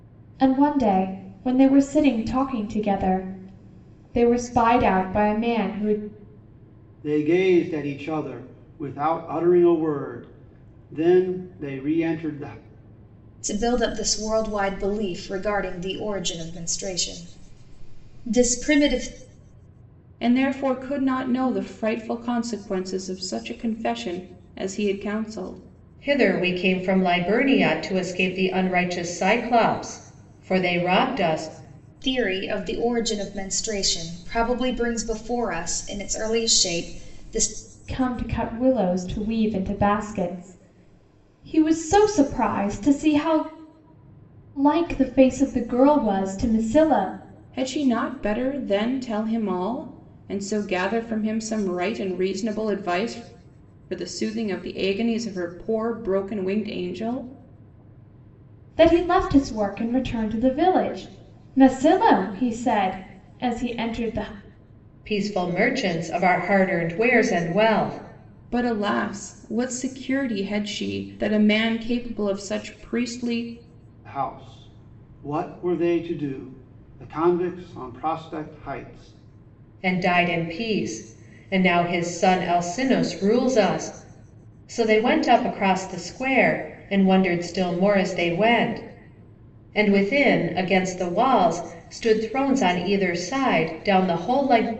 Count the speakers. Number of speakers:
5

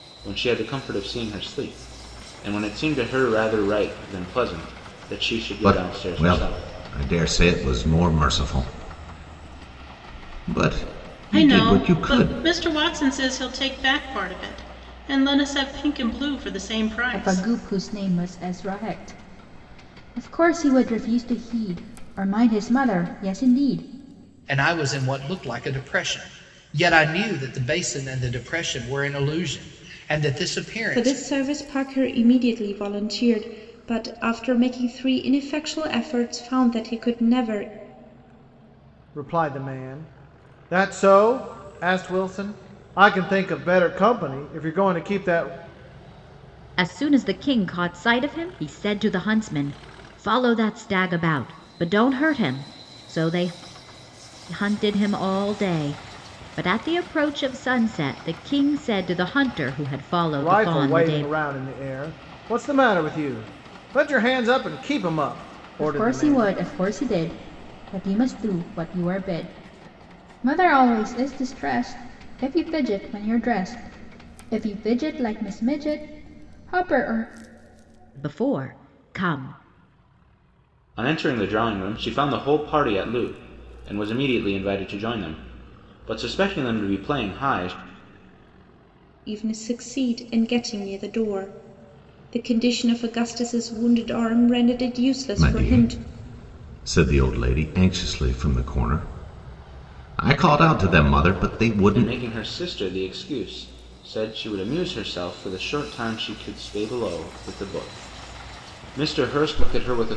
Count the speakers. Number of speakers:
8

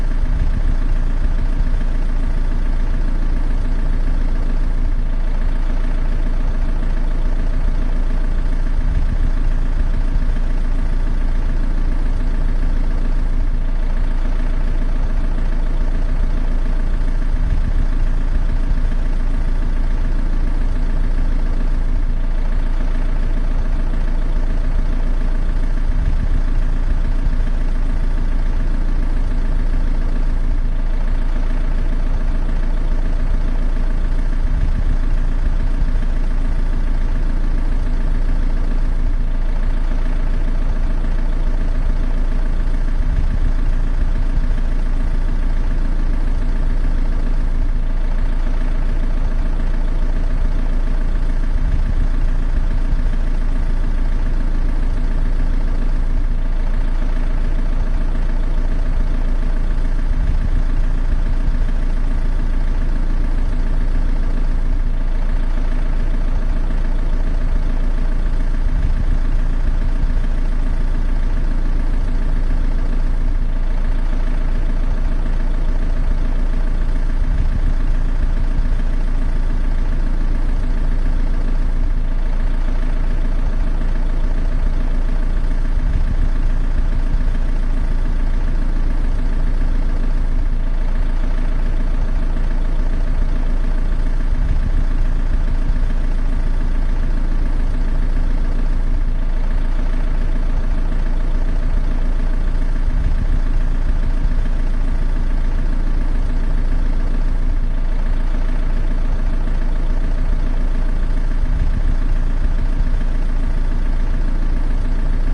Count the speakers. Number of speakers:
0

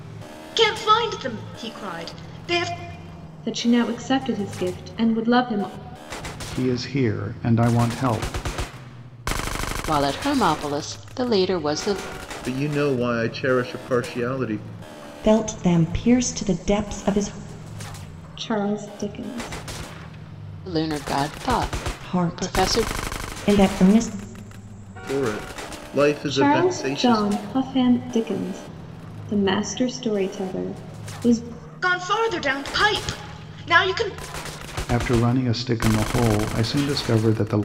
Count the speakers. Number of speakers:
6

